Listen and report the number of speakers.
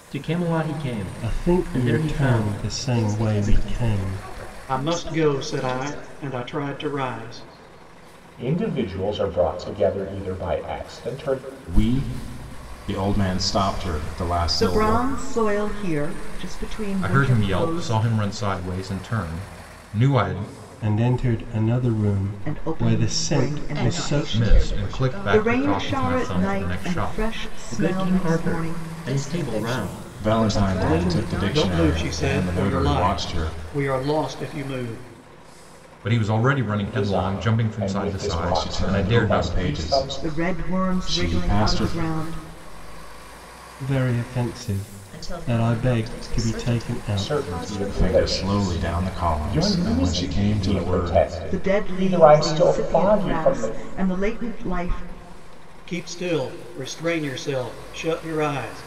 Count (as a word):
eight